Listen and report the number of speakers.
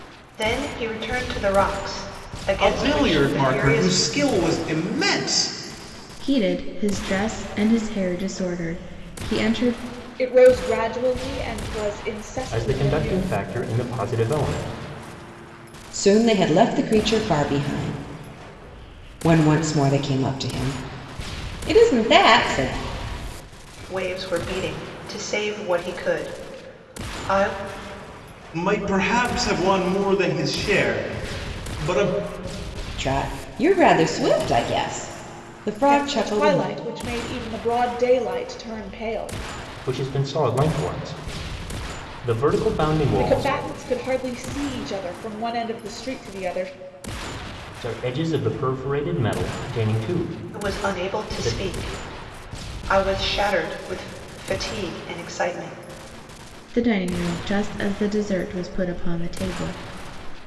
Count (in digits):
6